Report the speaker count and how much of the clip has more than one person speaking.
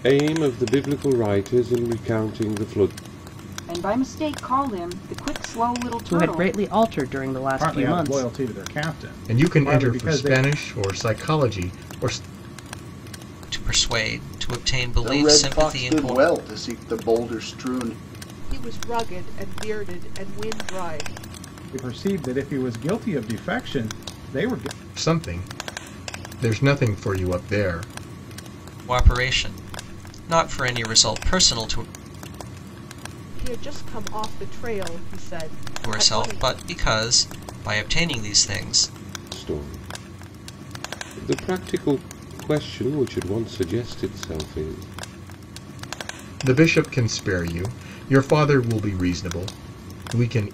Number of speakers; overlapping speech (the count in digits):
8, about 9%